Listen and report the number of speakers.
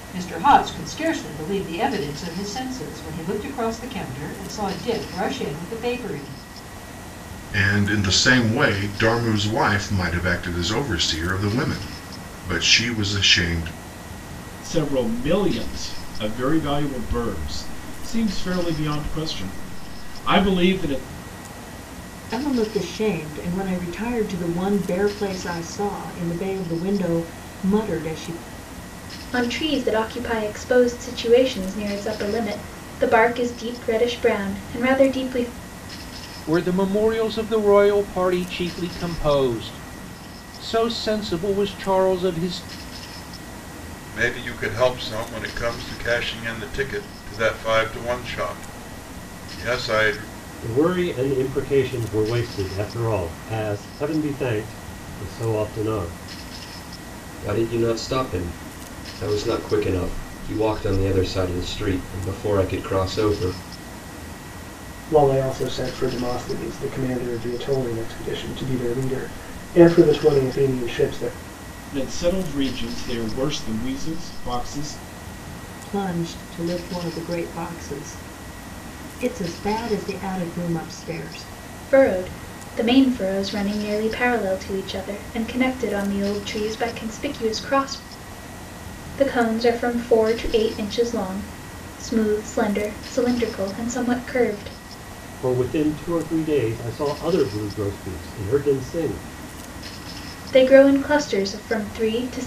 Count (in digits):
10